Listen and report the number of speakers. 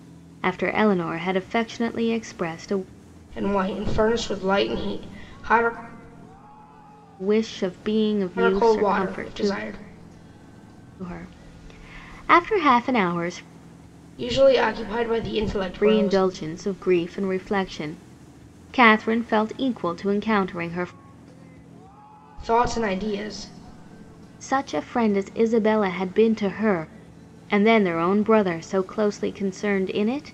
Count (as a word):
two